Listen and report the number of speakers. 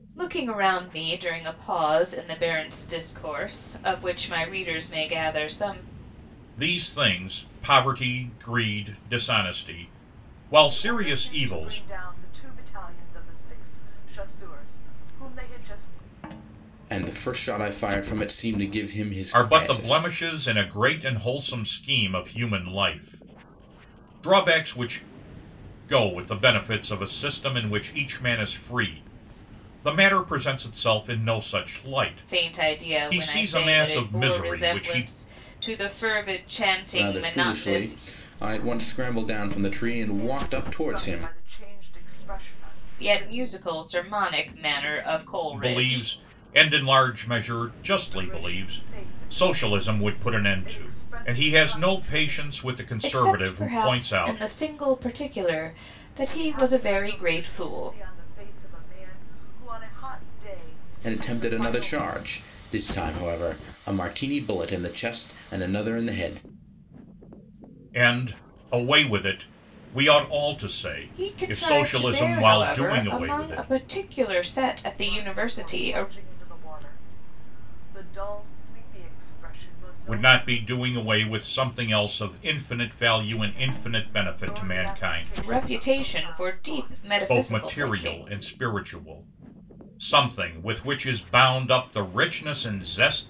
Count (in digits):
4